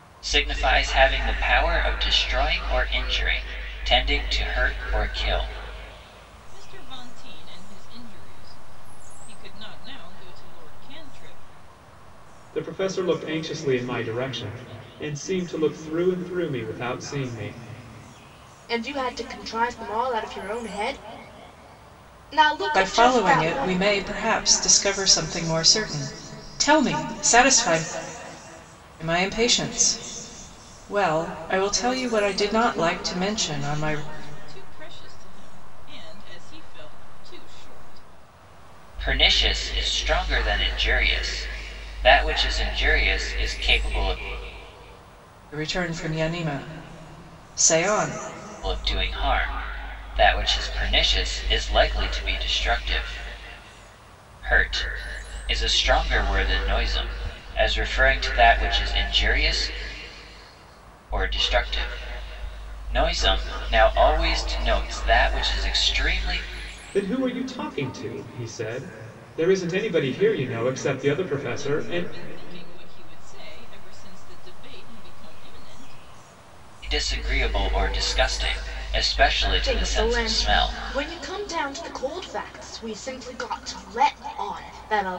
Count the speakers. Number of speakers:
5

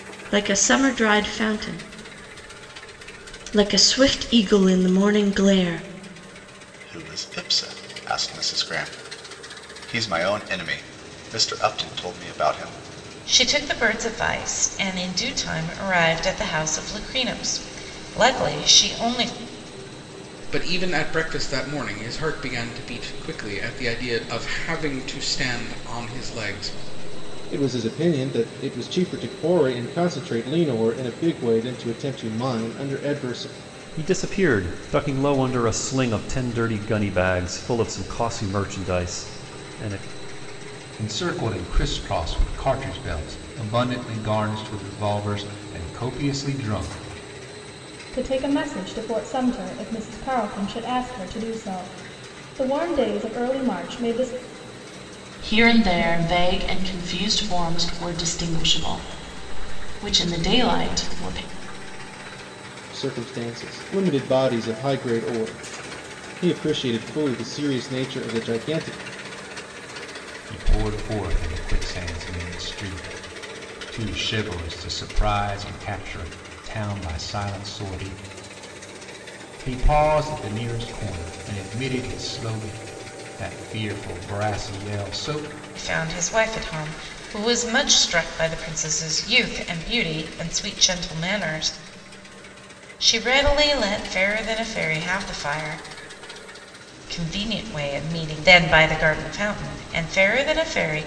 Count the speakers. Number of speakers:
9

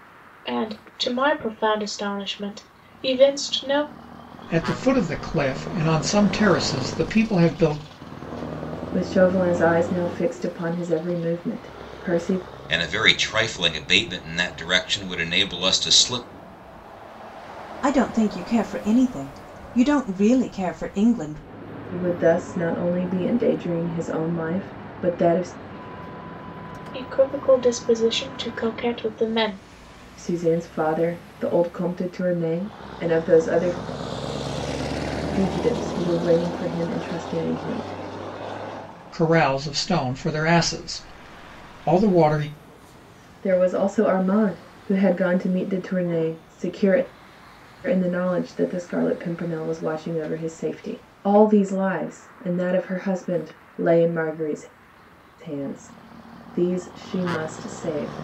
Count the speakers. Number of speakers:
5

